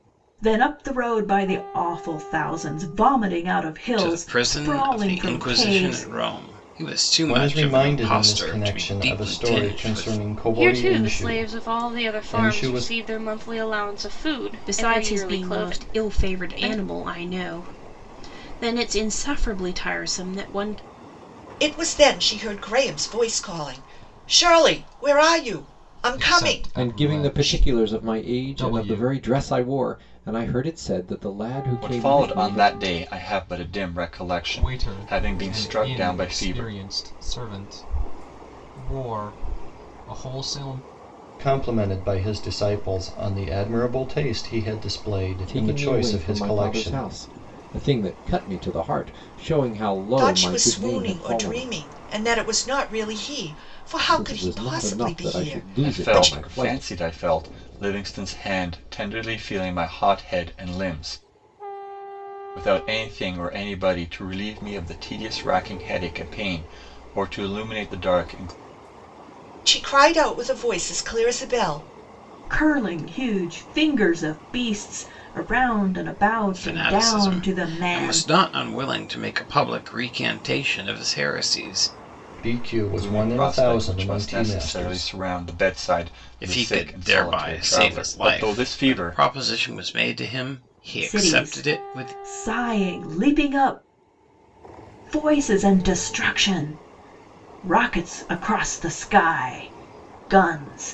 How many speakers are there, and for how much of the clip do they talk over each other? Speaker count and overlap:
nine, about 30%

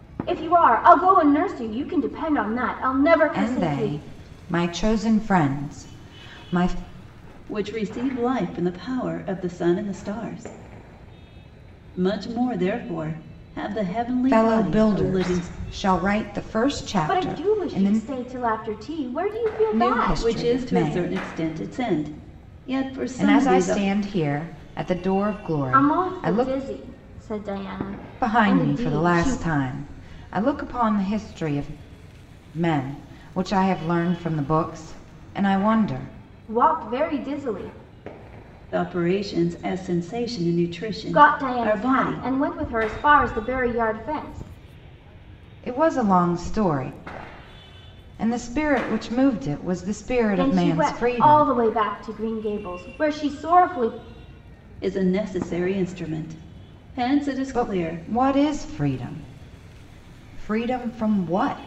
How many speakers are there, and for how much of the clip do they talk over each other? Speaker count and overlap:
three, about 17%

